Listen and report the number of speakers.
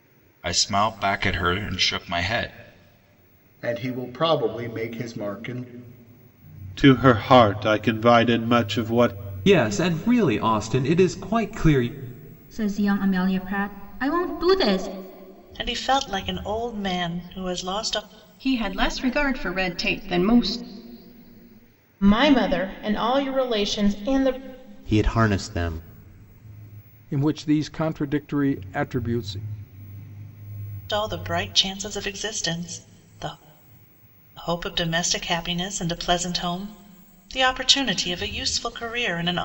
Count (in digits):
10